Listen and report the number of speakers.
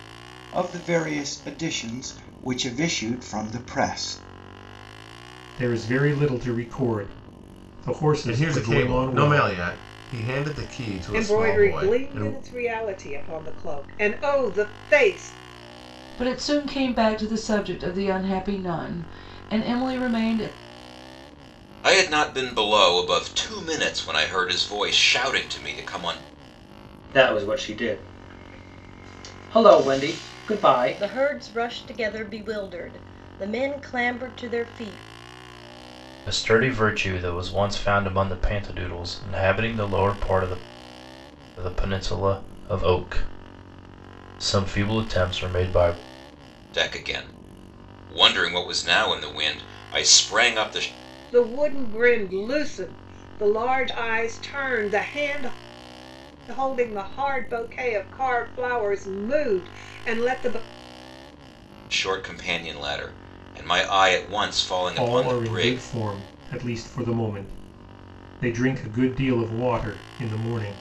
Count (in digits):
9